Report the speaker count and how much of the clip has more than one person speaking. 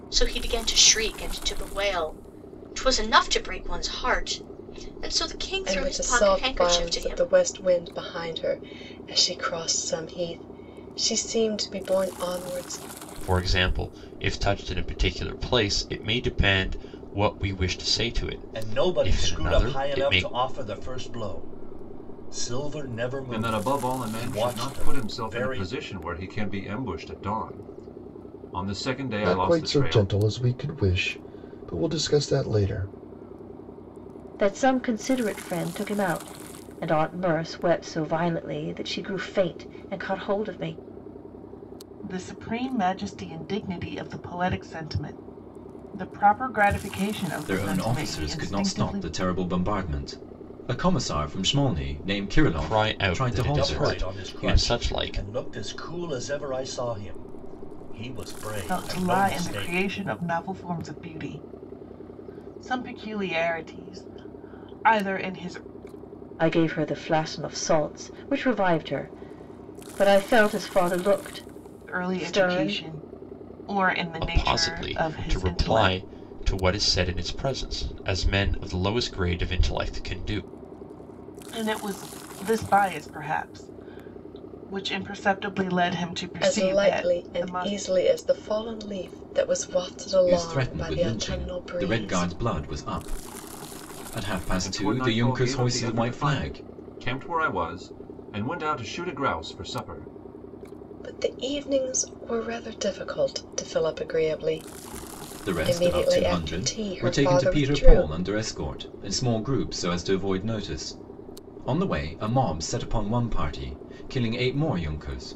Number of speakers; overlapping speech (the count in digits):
9, about 21%